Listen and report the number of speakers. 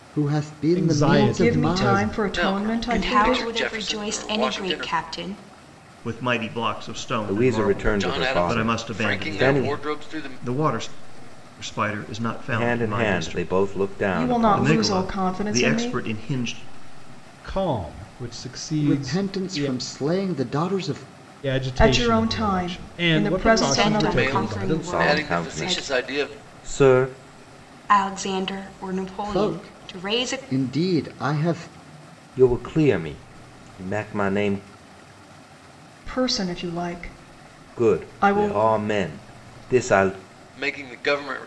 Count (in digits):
7